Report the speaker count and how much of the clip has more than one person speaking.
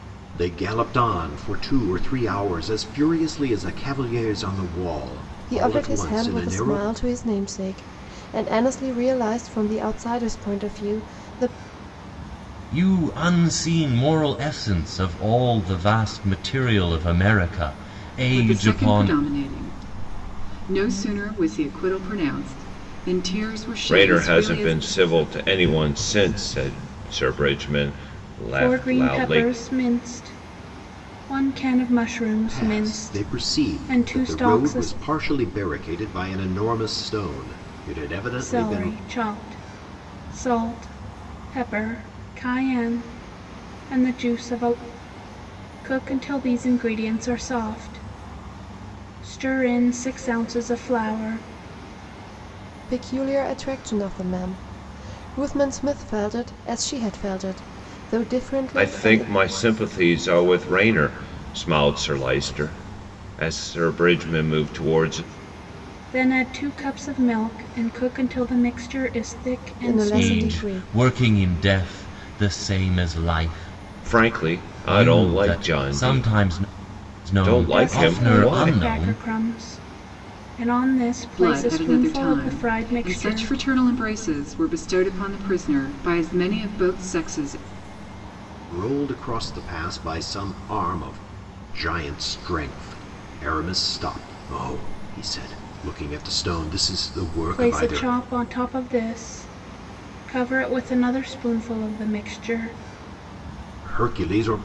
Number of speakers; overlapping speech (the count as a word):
six, about 16%